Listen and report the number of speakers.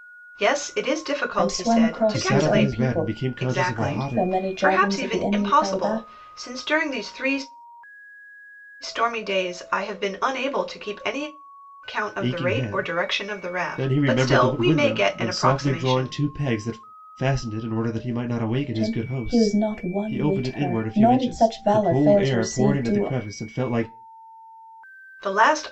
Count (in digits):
3